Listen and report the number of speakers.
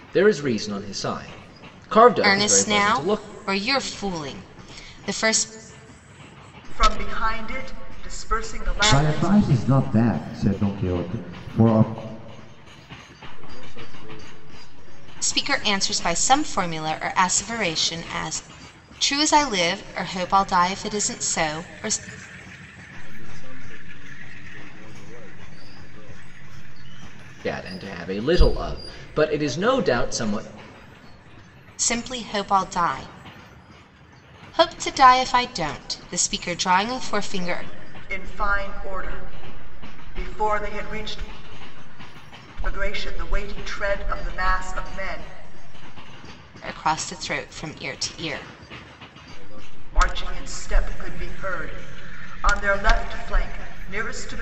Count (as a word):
five